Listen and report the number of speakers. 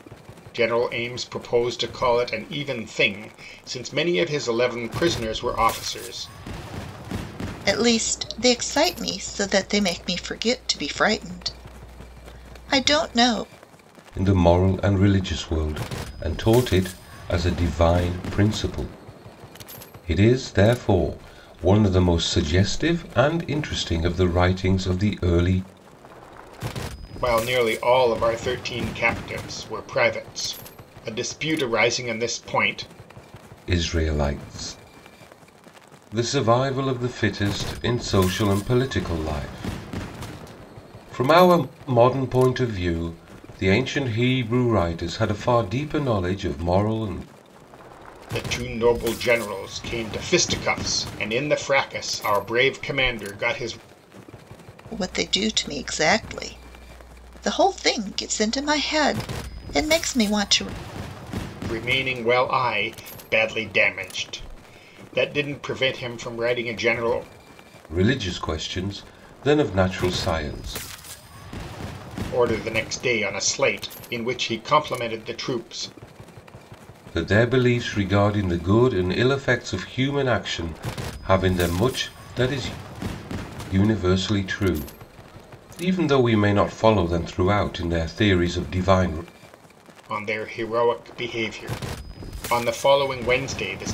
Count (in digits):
3